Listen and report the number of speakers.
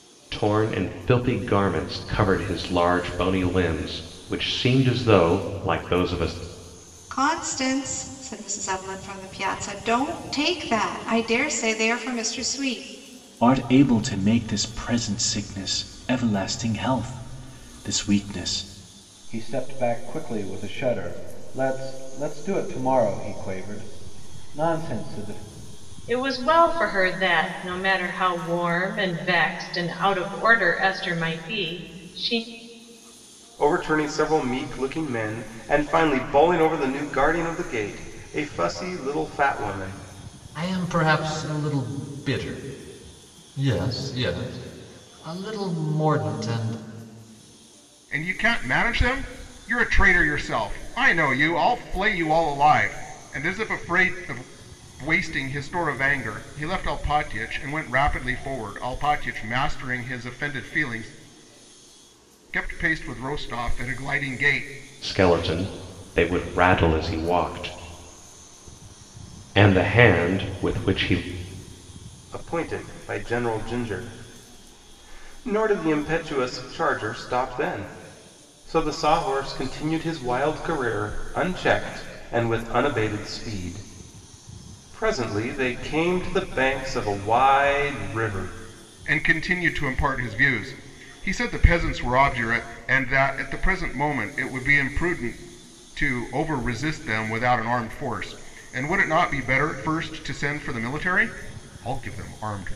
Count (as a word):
eight